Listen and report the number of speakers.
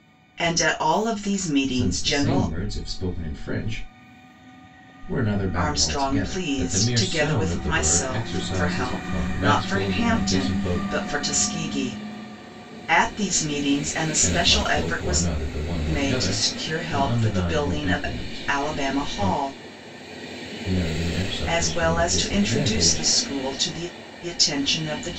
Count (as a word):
two